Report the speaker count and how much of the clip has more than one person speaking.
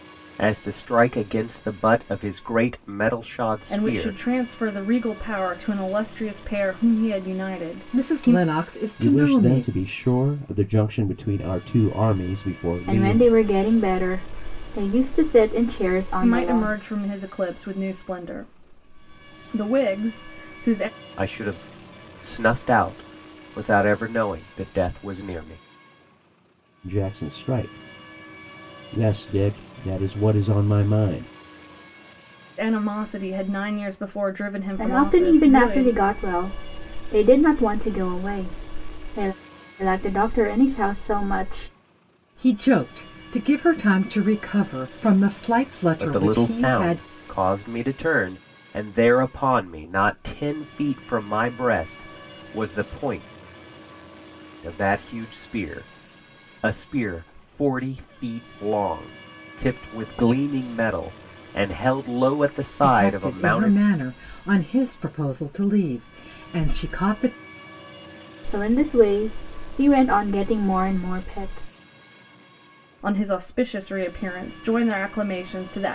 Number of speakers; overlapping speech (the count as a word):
five, about 8%